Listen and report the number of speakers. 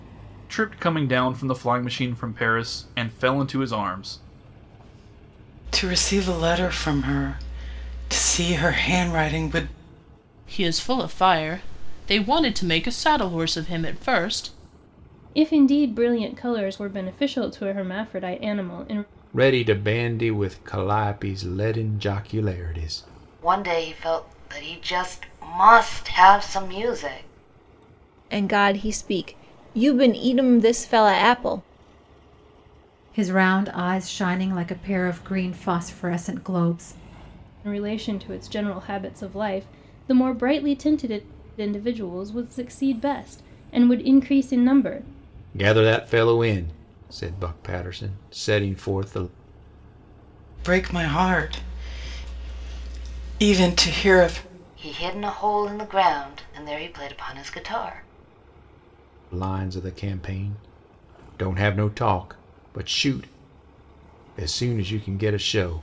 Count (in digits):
8